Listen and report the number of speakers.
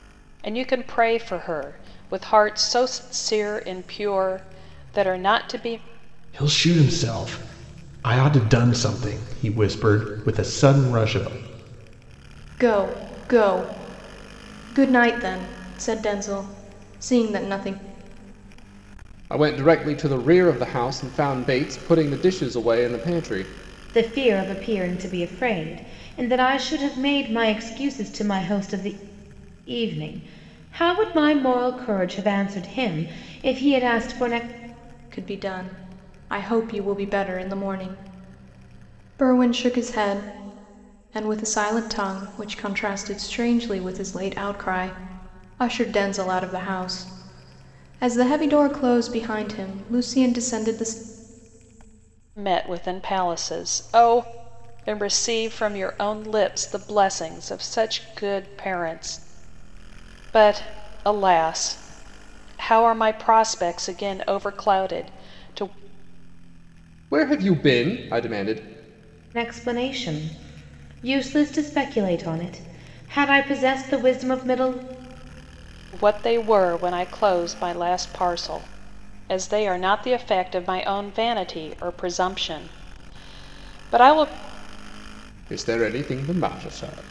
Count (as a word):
five